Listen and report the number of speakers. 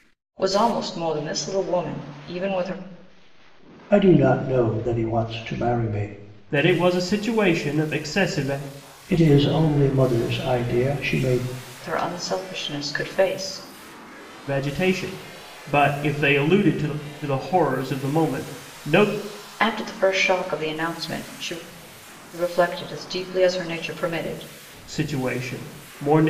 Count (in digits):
3